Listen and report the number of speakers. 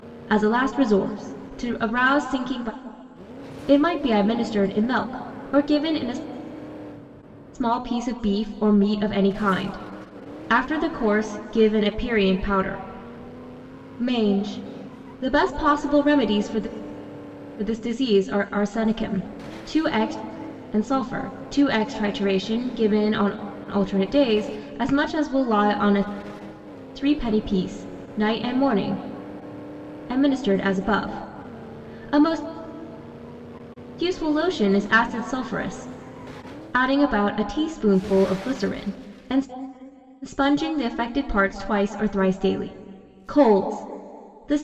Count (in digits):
1